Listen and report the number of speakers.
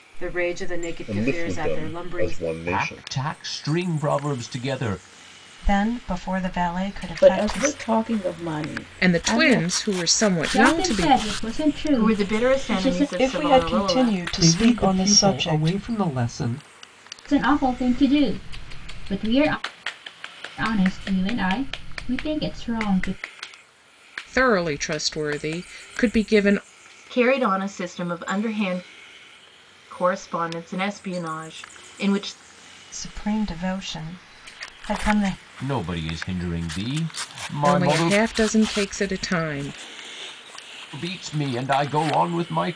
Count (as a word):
ten